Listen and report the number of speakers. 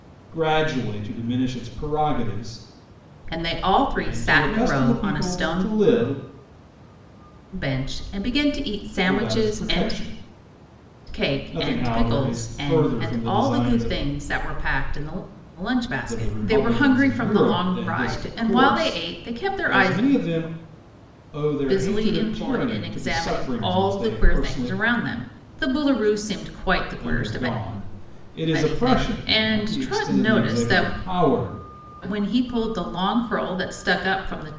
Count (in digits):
2